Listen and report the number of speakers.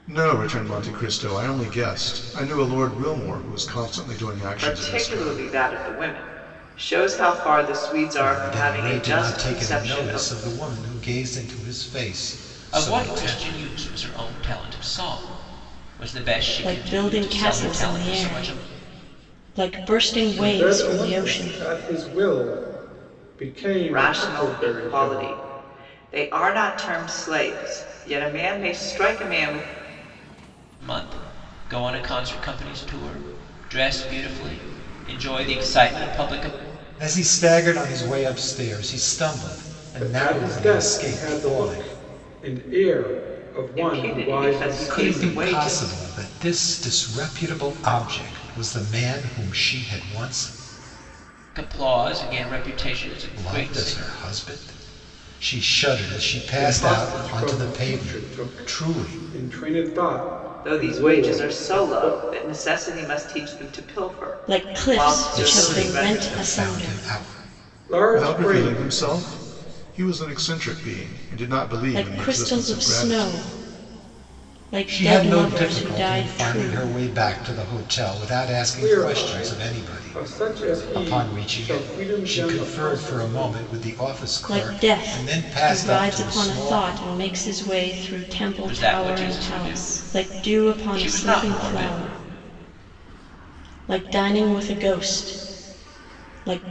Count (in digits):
6